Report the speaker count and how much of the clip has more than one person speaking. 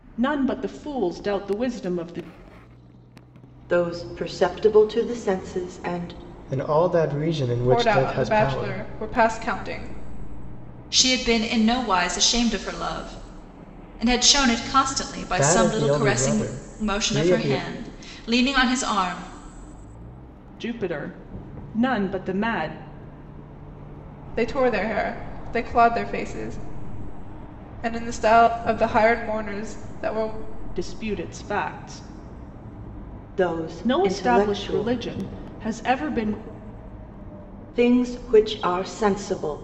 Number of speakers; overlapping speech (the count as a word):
five, about 11%